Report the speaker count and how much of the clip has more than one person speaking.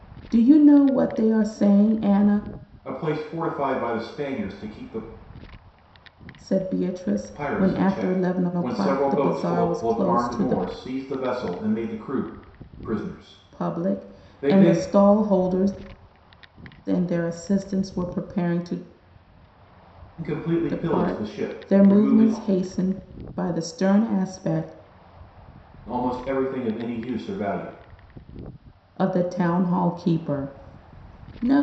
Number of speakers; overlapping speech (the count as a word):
two, about 20%